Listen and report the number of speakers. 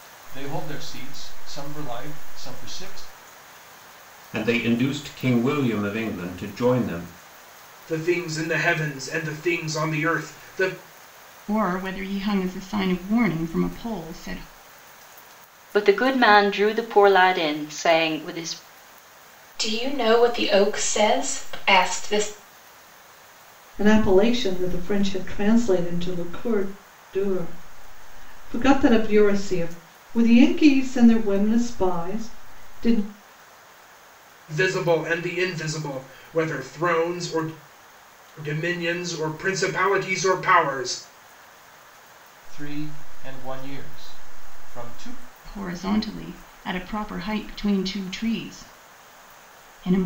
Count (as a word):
seven